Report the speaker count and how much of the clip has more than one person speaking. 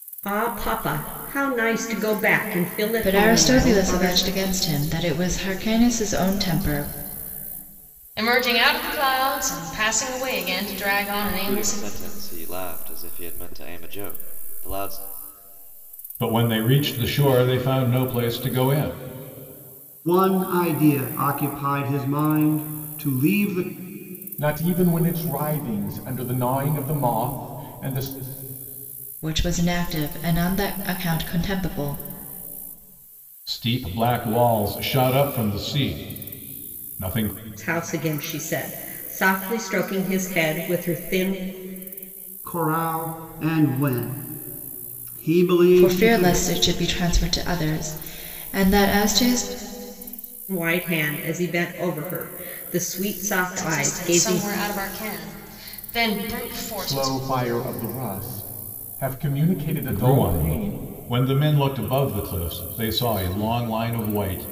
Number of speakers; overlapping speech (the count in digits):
7, about 8%